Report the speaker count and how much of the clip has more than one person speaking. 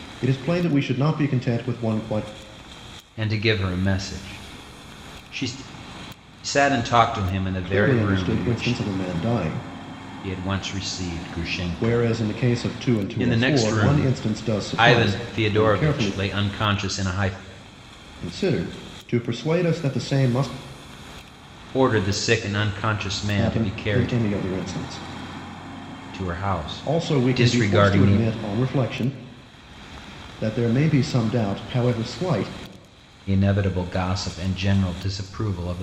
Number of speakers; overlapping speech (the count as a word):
two, about 19%